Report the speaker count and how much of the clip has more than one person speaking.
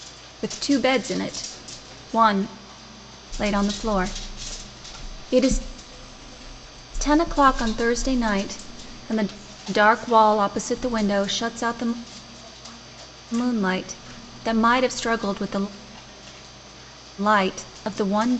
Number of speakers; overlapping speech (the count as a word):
one, no overlap